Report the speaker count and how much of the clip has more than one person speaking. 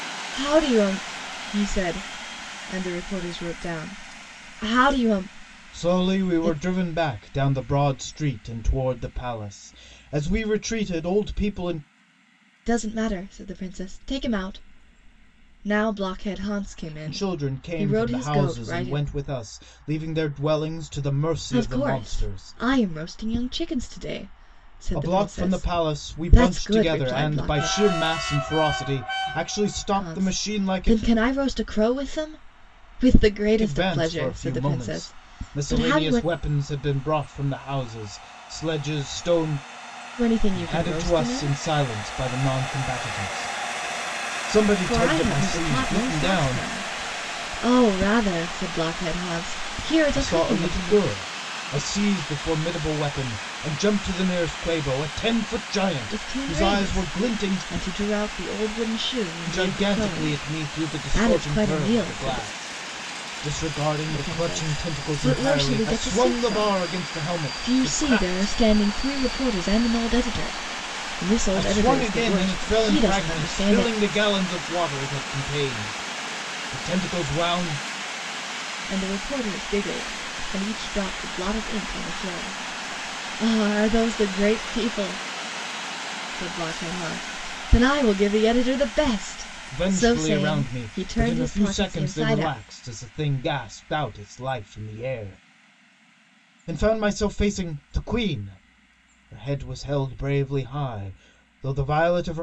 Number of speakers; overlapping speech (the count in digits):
2, about 27%